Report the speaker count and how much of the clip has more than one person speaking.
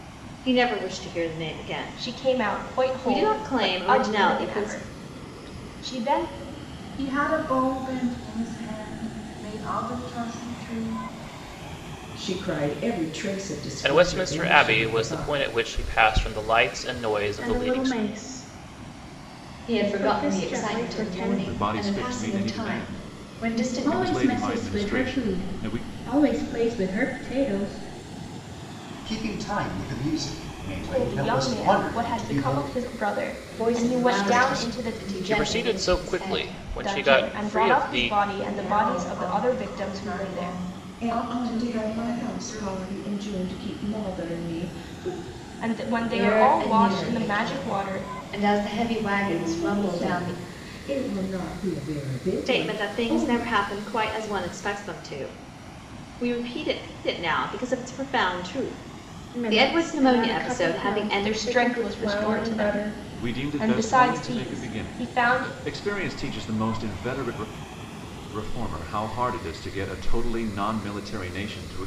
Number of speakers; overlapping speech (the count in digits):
10, about 45%